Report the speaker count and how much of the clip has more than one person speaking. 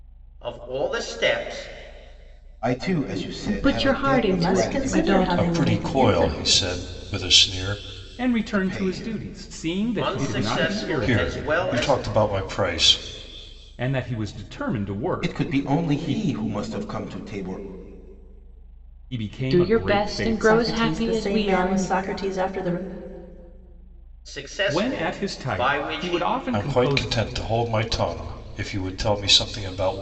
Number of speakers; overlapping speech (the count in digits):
6, about 41%